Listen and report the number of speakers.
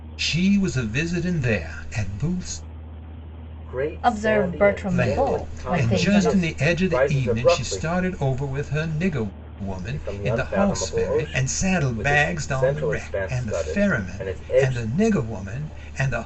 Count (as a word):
three